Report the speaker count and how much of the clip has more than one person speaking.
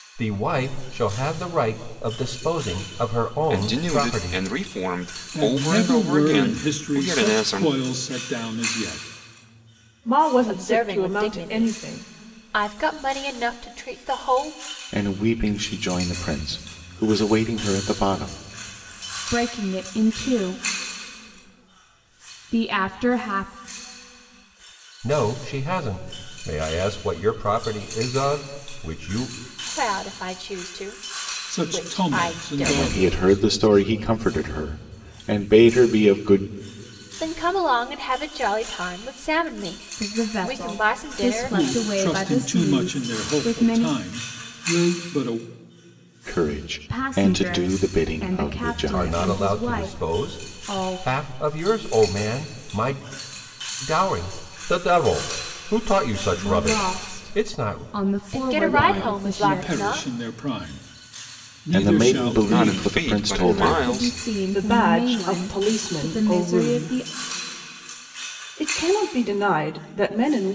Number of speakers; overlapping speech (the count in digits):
7, about 34%